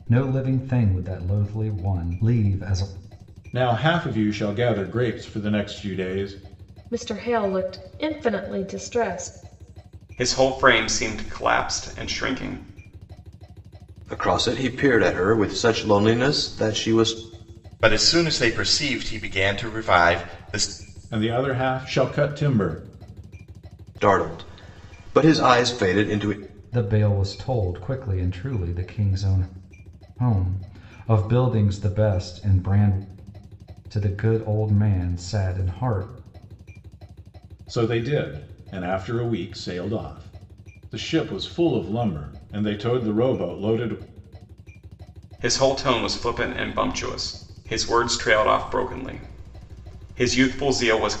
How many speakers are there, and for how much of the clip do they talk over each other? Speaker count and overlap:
six, no overlap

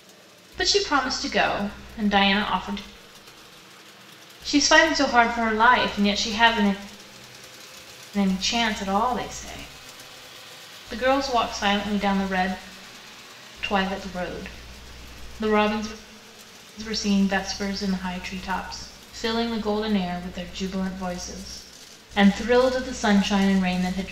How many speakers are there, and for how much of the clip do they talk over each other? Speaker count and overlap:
one, no overlap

